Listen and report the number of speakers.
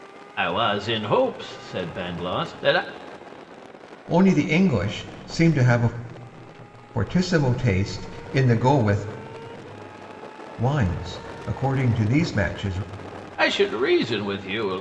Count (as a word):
two